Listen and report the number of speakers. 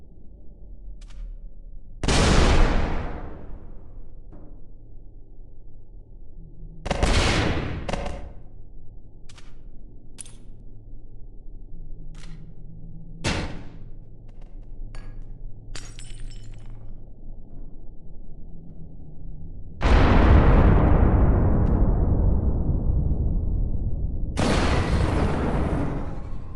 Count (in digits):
0